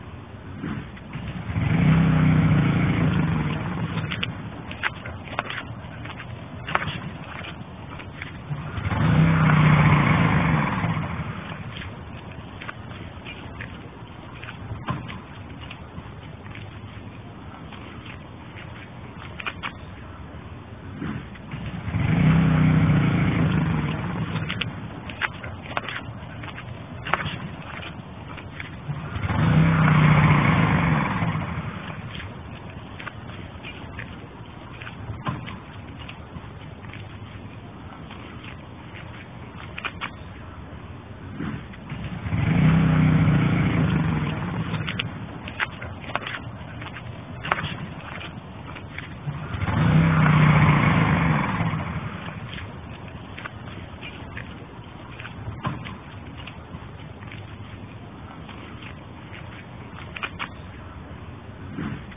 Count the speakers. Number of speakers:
zero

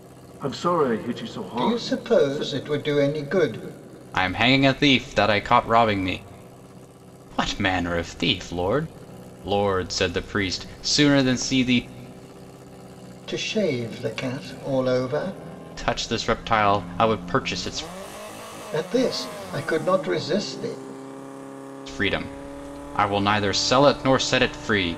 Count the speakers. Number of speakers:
three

